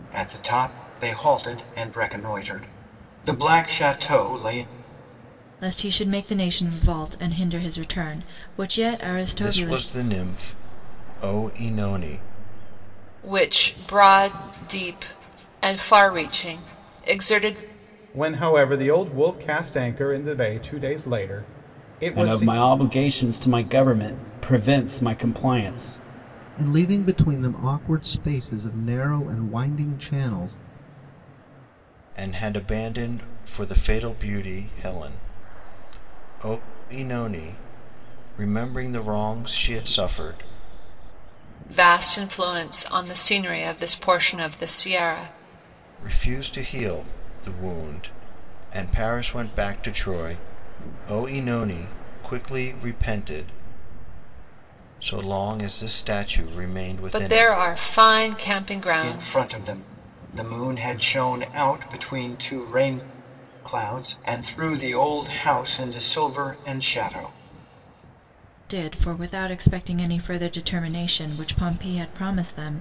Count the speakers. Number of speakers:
seven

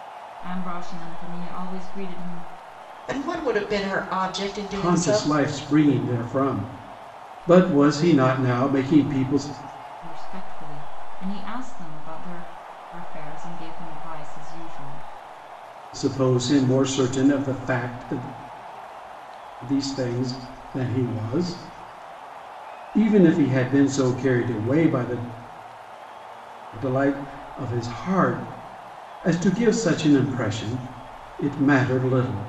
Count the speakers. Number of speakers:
three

